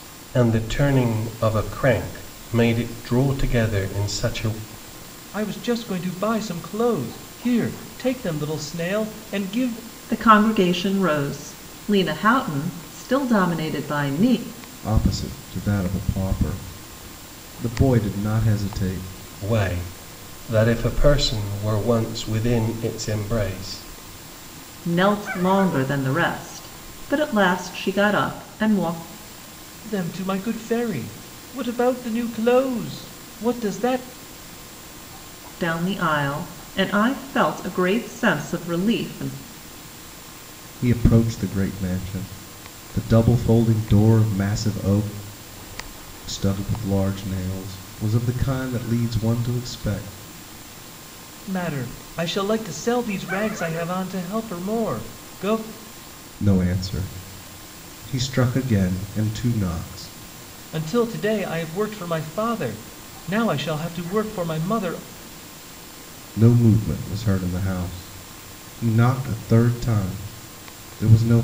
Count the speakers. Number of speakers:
four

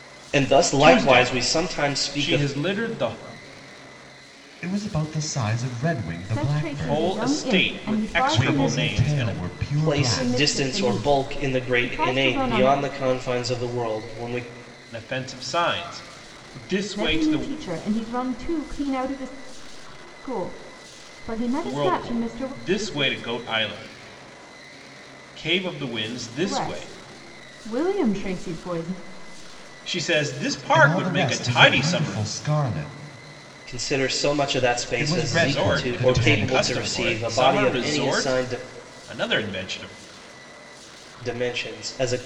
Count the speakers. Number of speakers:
four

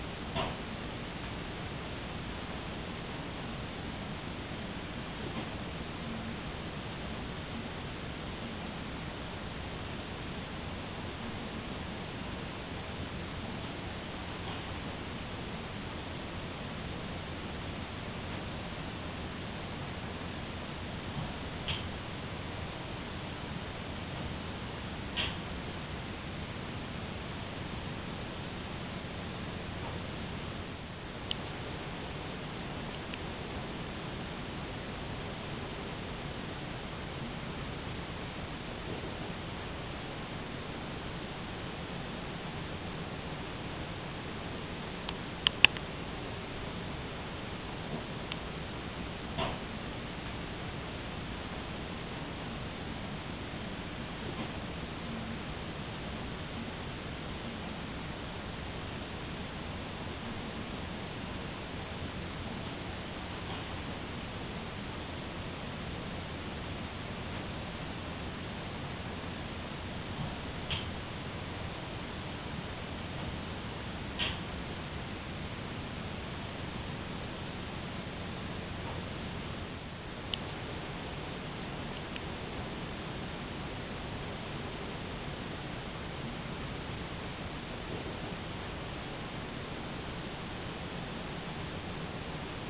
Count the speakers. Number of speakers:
zero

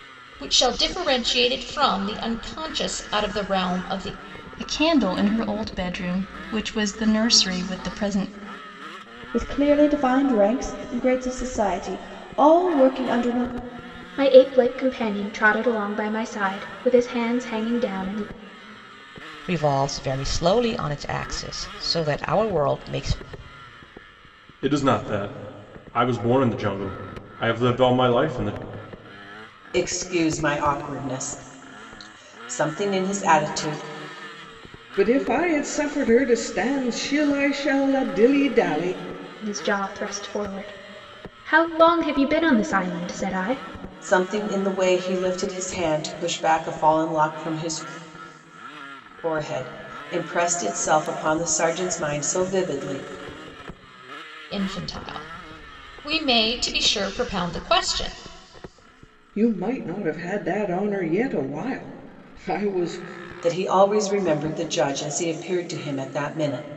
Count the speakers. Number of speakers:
eight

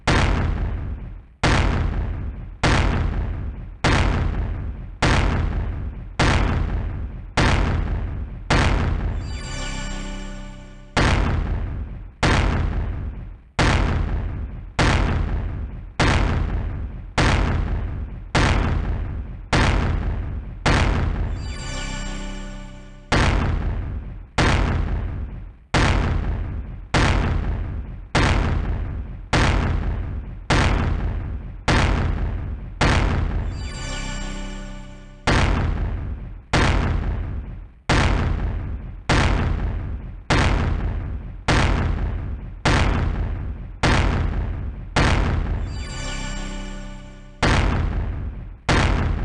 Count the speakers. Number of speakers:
zero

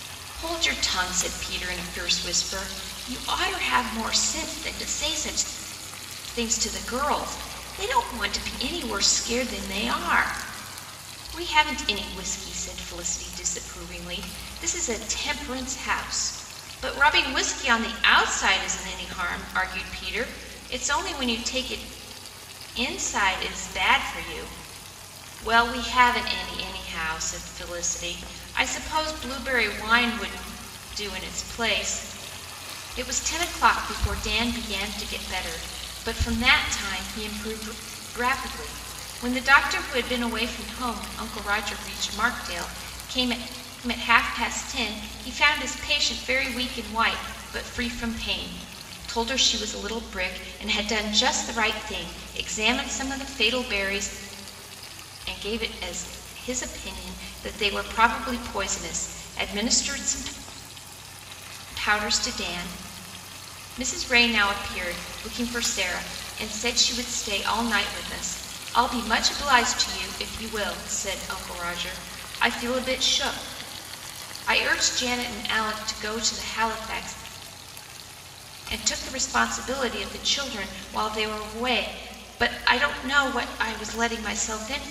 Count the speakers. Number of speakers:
one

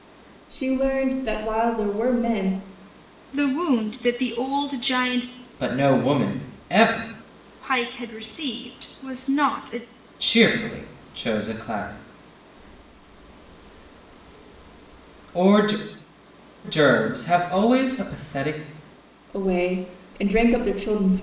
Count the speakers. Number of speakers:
three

